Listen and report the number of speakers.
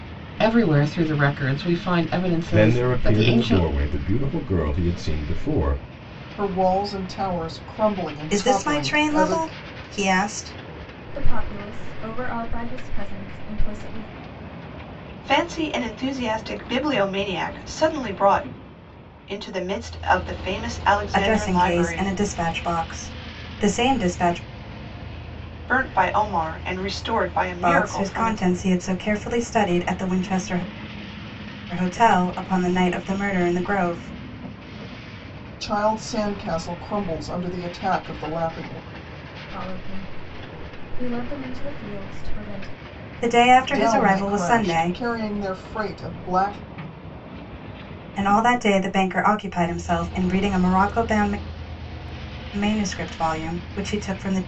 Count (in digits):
6